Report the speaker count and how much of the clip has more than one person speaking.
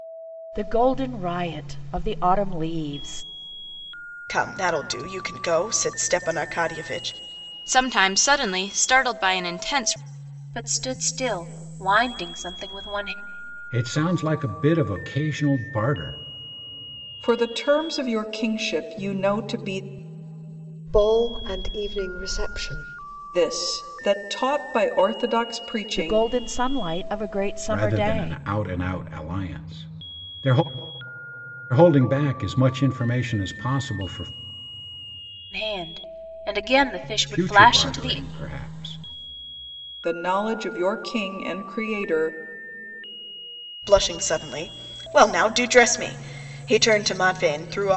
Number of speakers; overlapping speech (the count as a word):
seven, about 4%